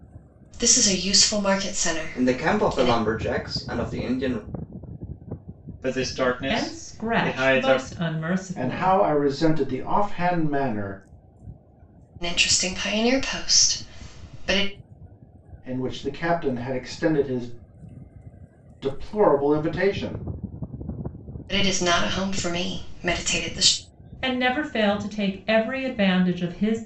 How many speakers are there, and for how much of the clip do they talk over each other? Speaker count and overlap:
five, about 10%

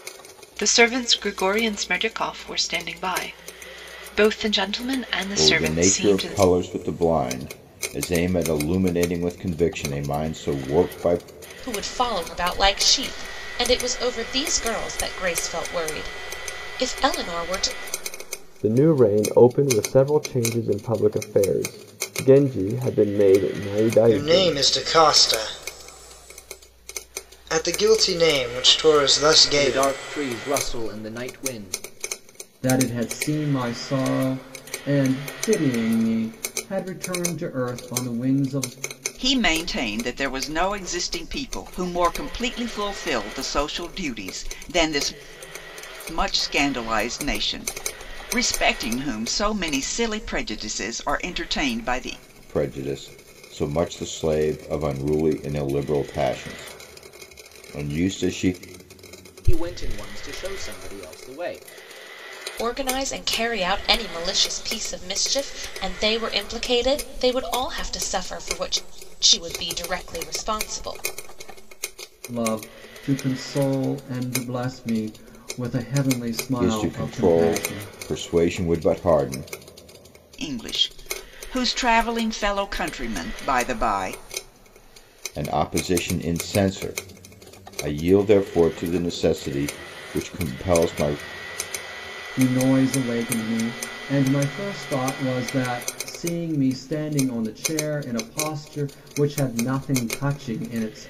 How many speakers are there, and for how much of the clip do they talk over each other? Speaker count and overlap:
eight, about 4%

